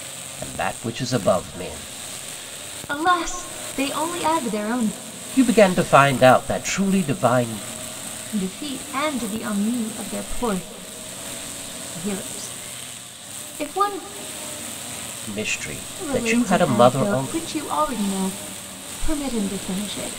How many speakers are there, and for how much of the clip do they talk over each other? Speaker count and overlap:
2, about 7%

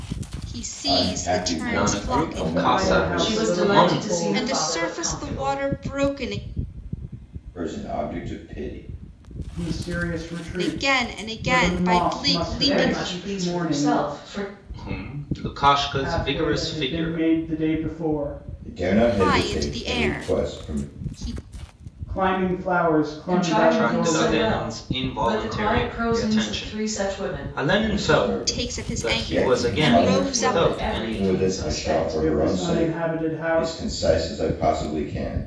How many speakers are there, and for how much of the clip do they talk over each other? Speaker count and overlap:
5, about 59%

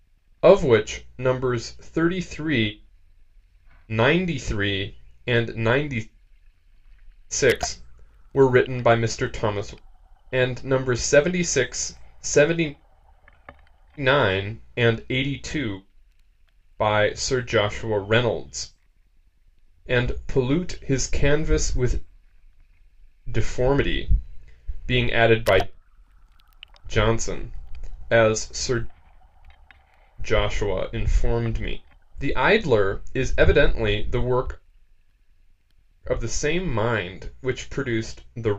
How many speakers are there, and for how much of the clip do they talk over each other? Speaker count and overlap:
1, no overlap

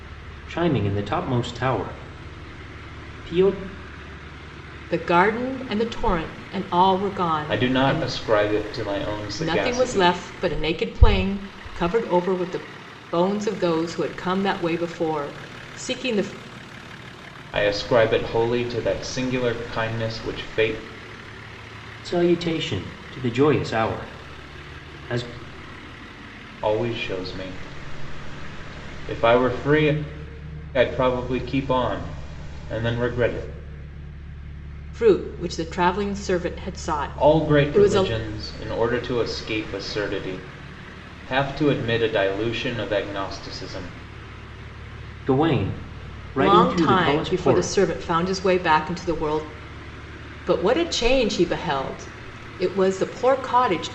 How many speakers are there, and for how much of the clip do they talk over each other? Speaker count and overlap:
3, about 7%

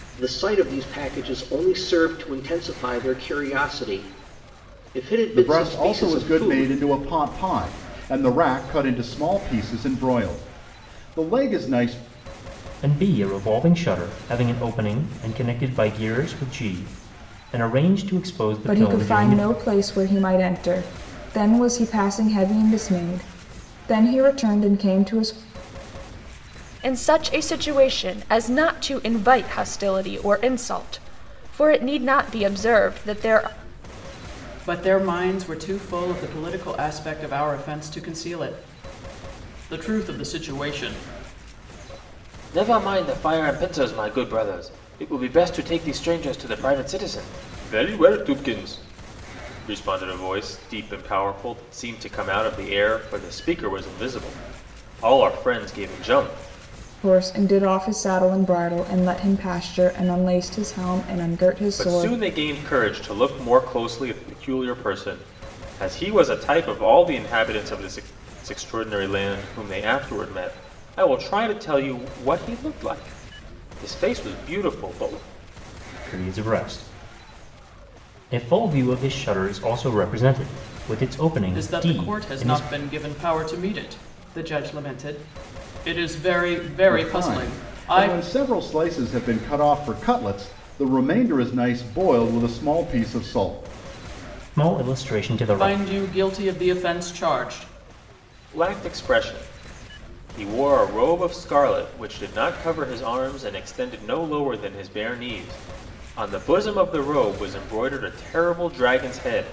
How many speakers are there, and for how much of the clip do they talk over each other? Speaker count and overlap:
7, about 5%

